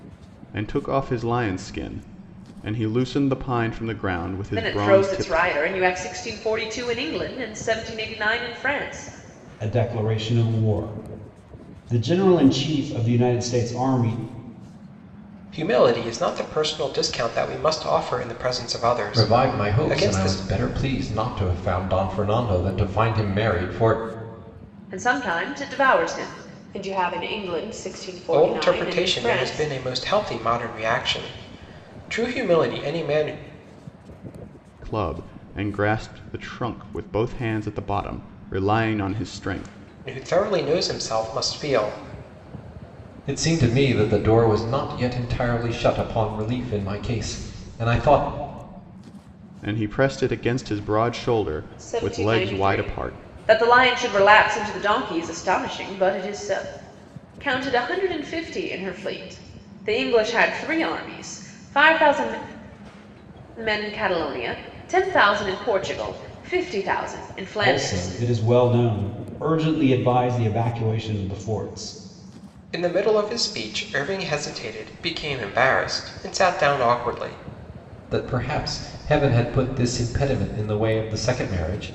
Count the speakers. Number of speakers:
5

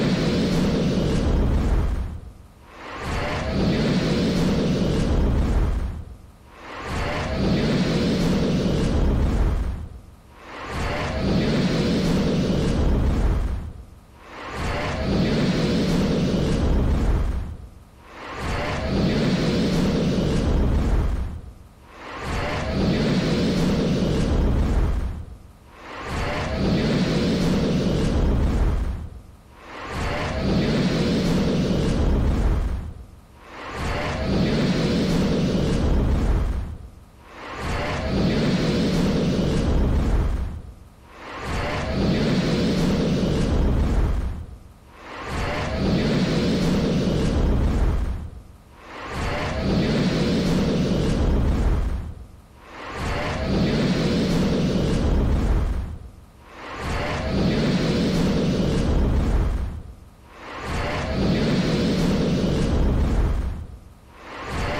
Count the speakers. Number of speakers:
0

